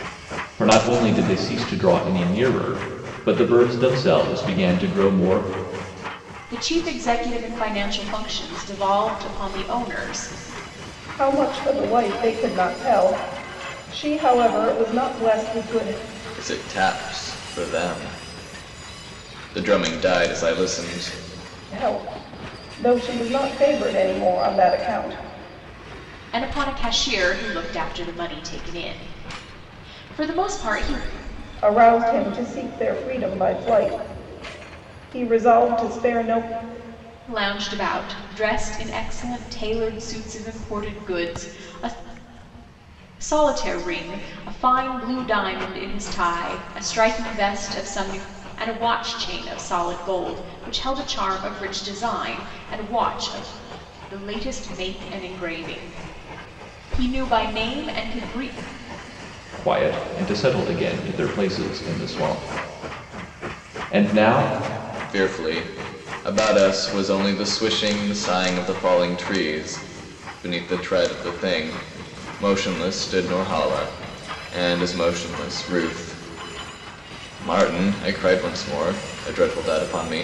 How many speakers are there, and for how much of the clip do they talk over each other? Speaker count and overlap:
4, no overlap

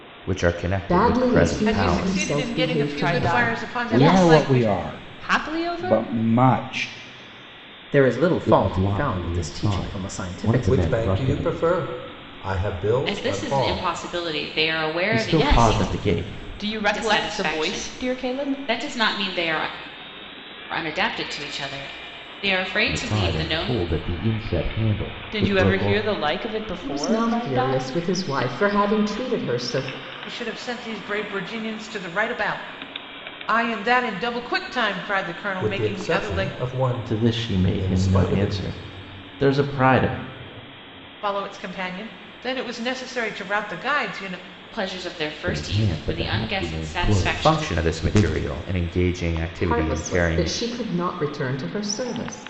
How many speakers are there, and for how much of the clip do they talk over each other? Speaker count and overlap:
10, about 41%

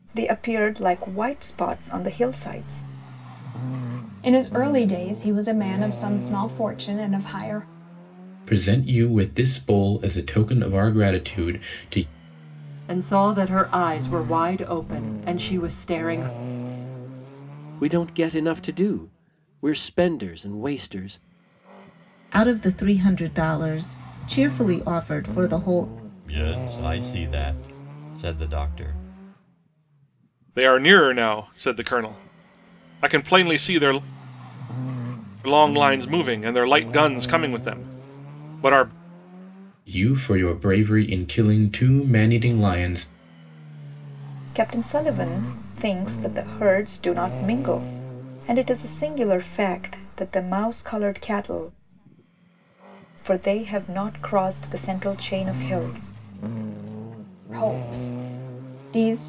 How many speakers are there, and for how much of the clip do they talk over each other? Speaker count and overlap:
8, no overlap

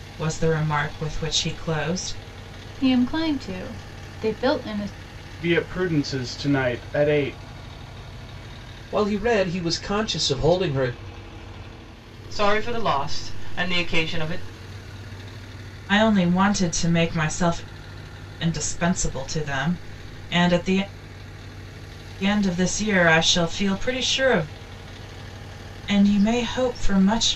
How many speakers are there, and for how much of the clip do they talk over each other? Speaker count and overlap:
5, no overlap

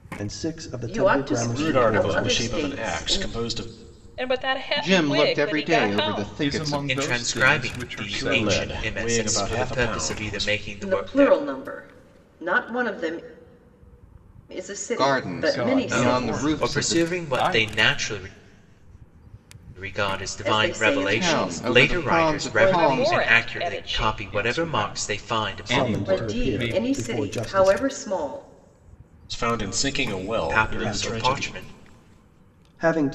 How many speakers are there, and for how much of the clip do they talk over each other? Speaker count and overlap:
7, about 61%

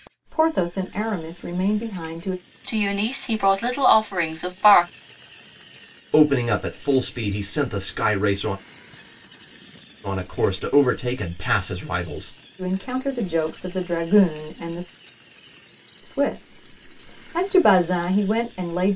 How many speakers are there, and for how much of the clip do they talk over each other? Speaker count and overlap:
3, no overlap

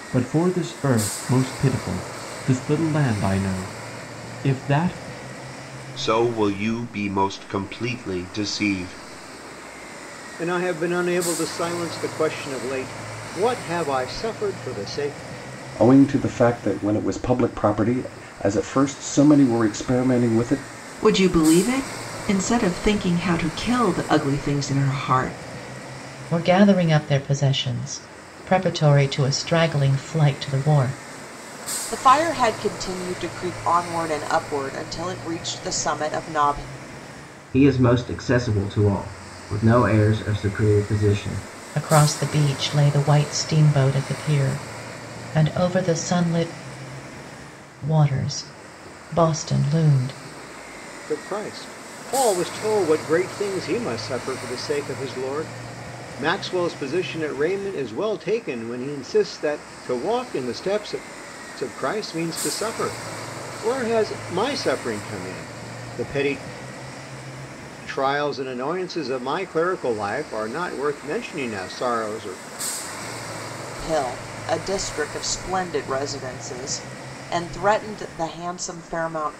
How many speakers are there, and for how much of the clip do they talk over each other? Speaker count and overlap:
8, no overlap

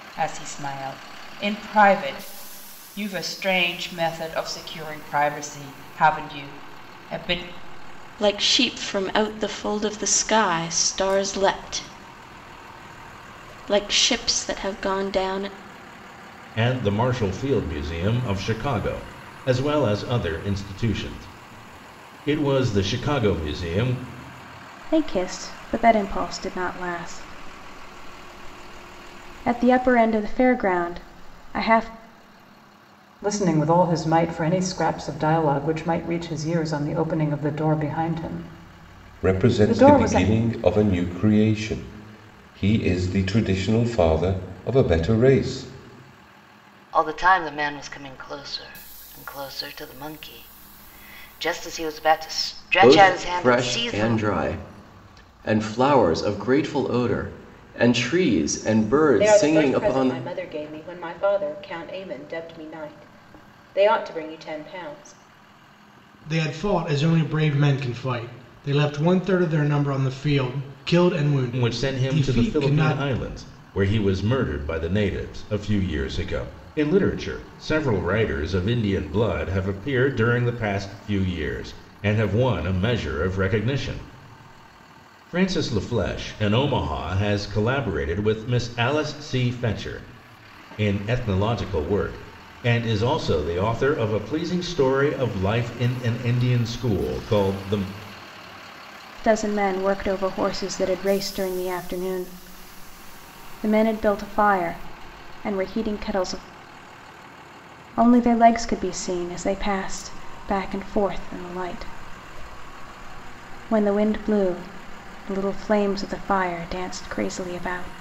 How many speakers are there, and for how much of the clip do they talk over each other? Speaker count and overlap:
10, about 4%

